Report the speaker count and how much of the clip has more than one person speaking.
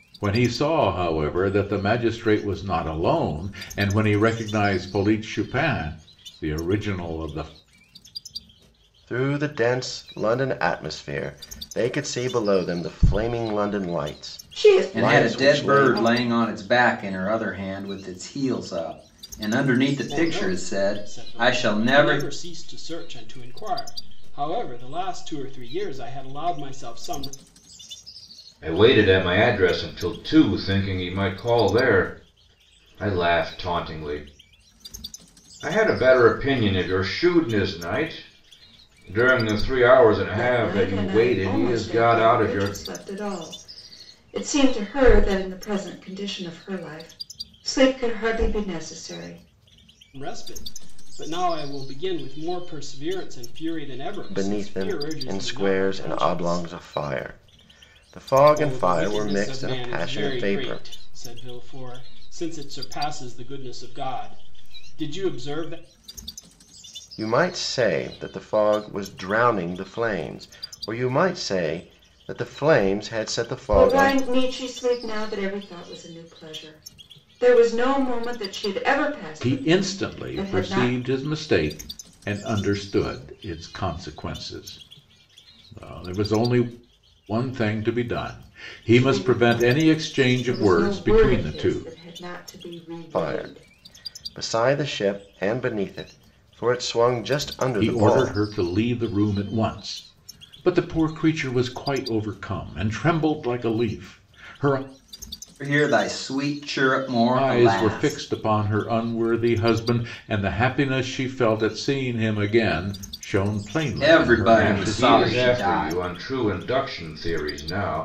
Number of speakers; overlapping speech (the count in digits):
6, about 17%